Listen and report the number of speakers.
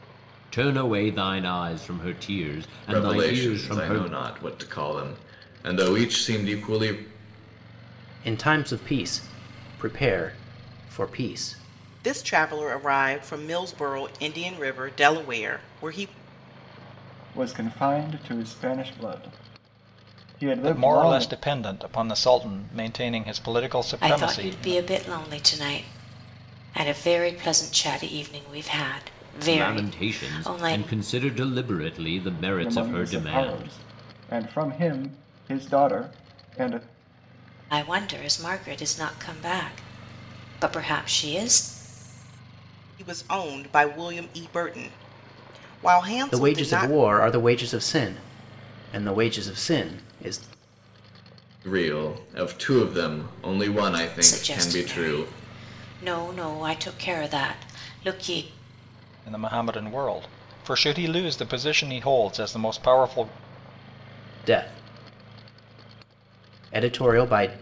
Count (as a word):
seven